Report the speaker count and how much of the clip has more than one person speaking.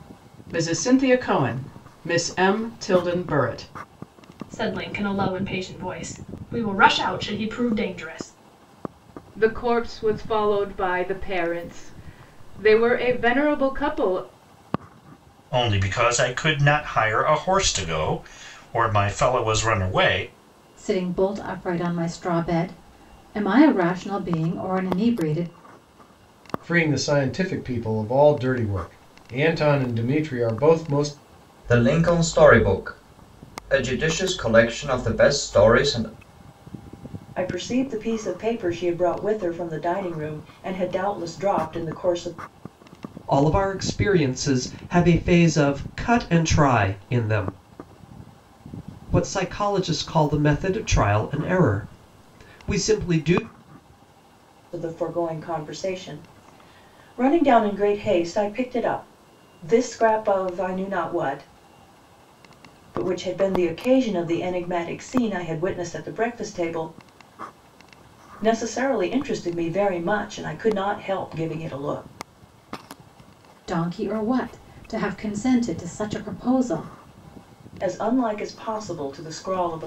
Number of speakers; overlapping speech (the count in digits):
9, no overlap